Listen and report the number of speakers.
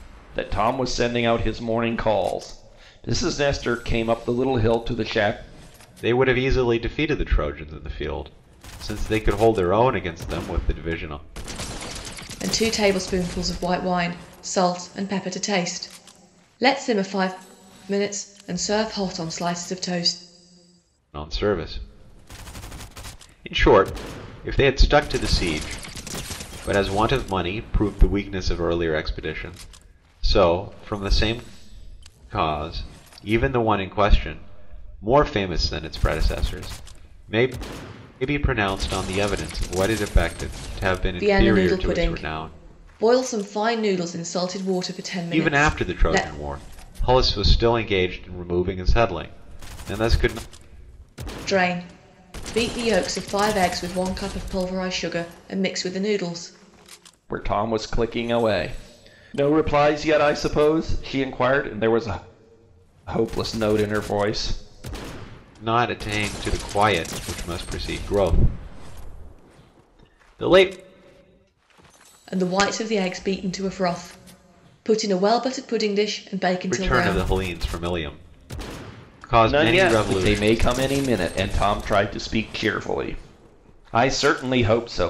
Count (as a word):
three